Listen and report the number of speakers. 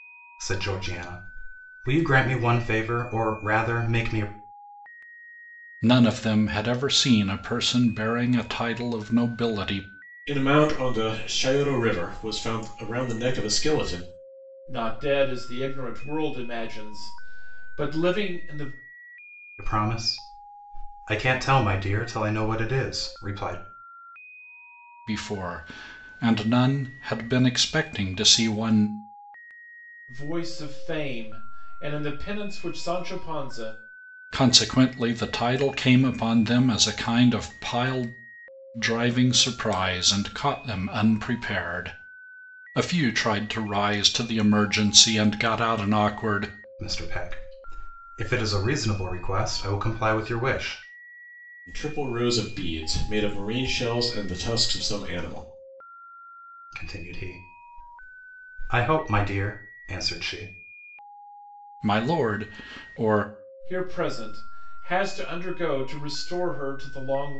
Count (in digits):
4